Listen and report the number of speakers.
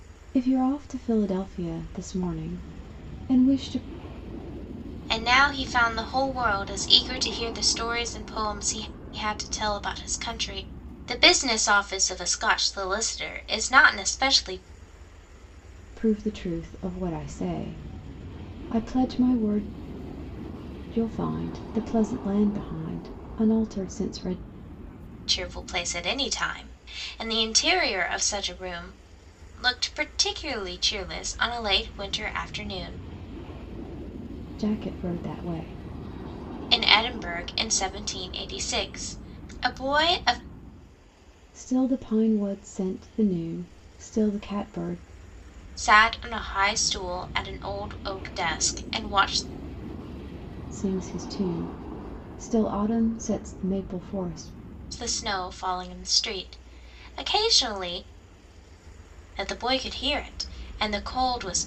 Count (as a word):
two